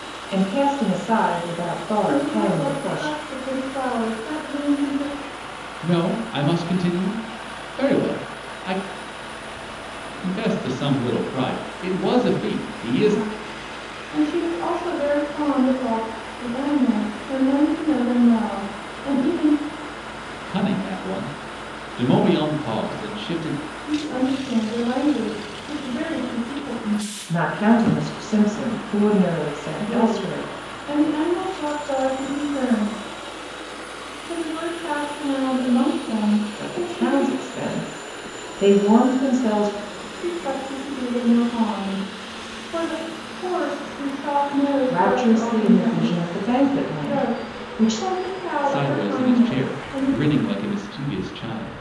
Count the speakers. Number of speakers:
three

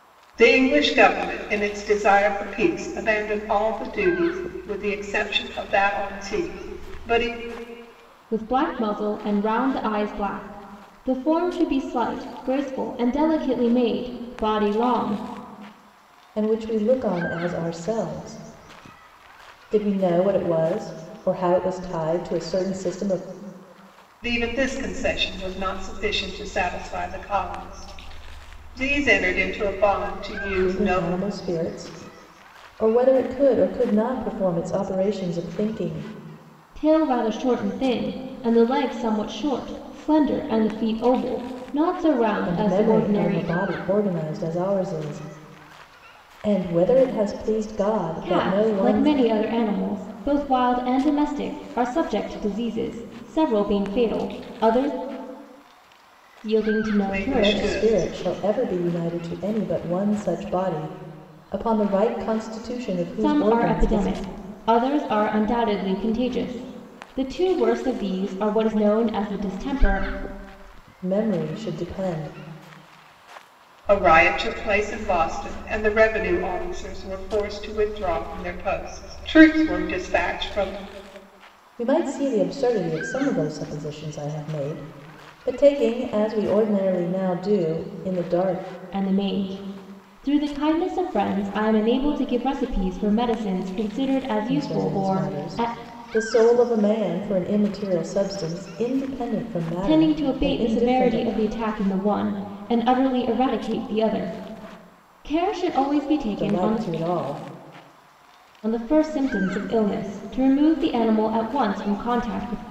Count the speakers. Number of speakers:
three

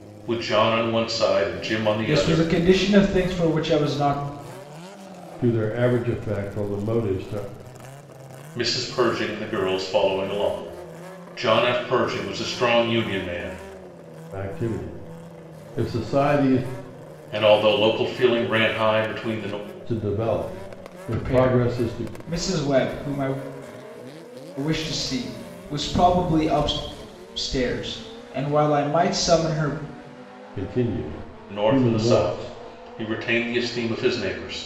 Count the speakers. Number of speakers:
three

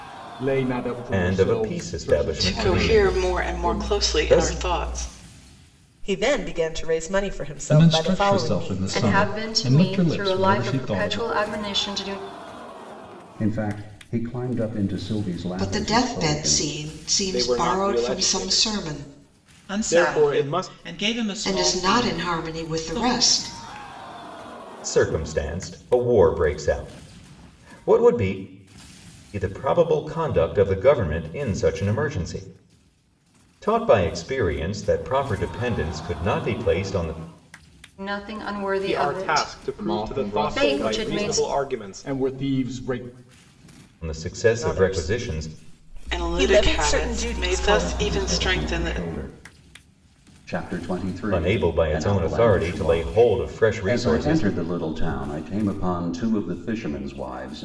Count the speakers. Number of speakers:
ten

